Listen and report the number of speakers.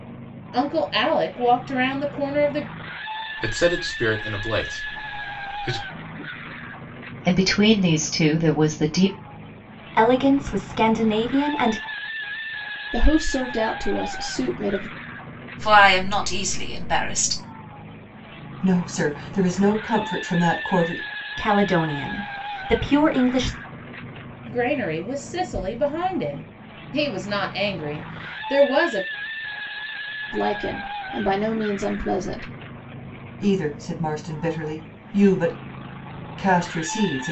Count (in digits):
7